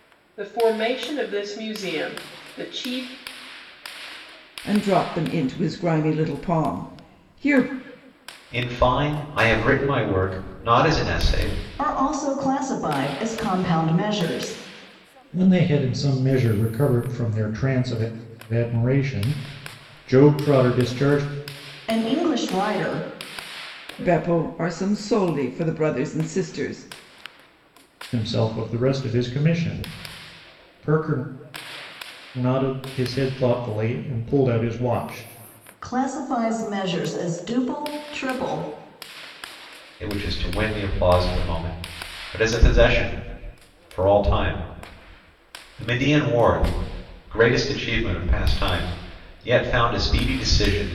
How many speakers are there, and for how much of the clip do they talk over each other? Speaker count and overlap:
five, no overlap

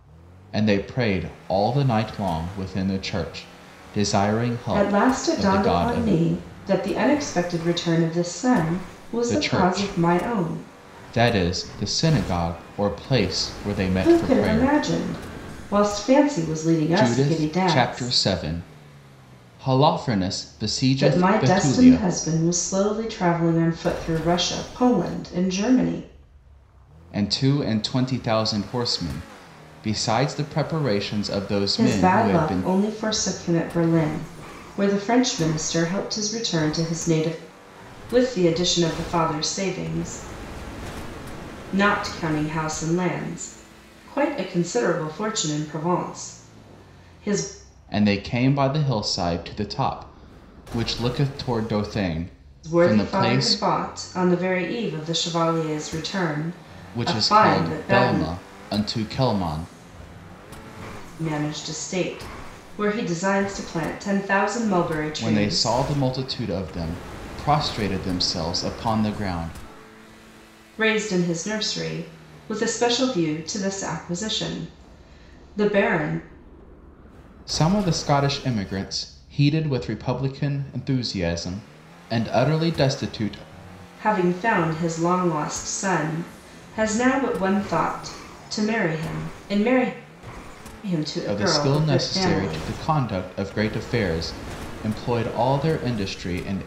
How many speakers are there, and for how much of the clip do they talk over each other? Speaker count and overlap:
two, about 12%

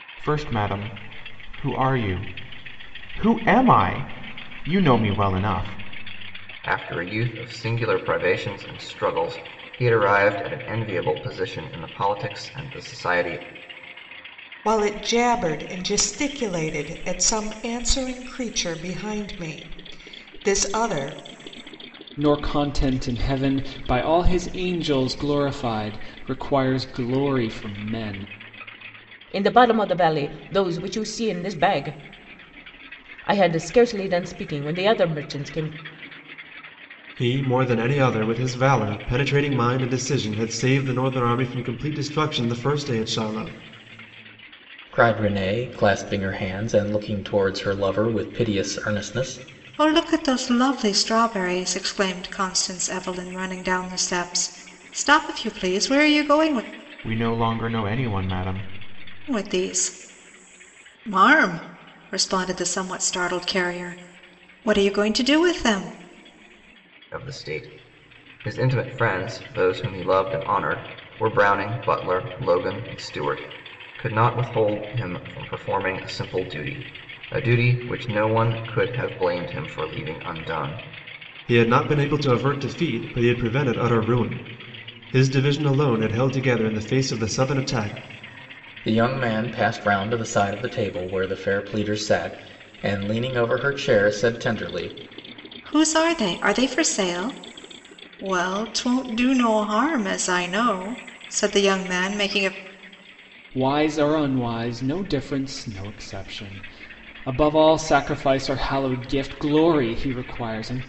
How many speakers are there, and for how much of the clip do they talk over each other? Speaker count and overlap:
eight, no overlap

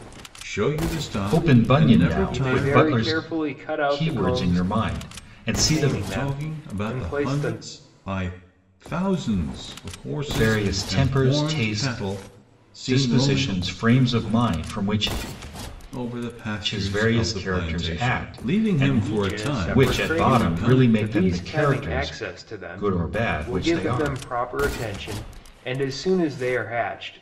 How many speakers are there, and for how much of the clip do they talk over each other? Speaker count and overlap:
three, about 53%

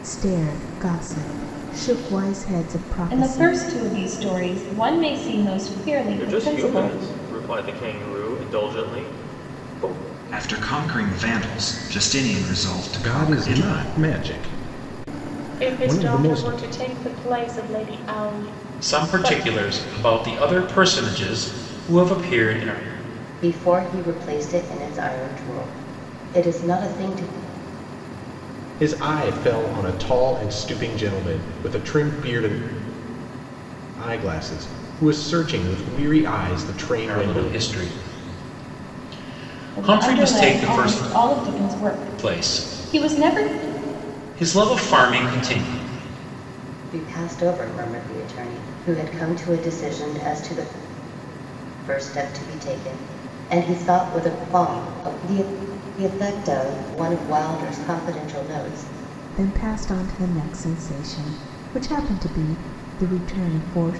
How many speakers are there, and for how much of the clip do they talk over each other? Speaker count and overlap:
nine, about 11%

